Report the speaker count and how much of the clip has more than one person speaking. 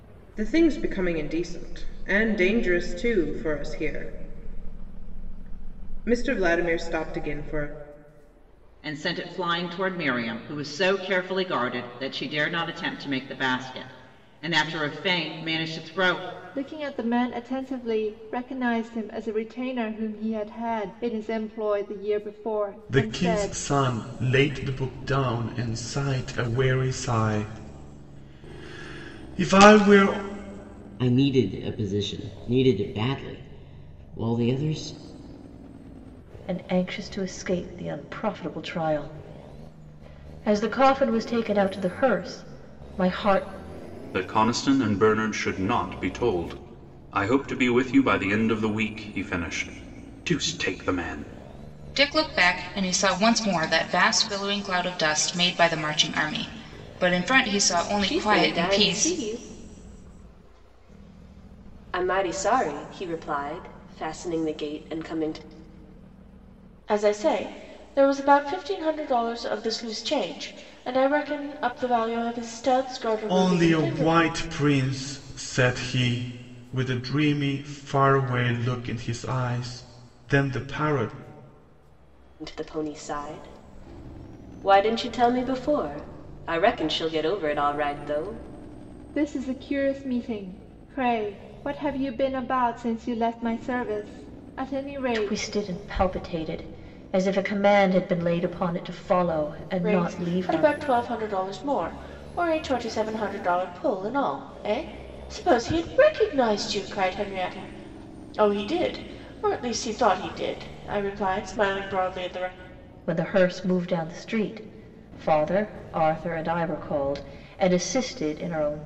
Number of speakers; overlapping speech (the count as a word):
ten, about 3%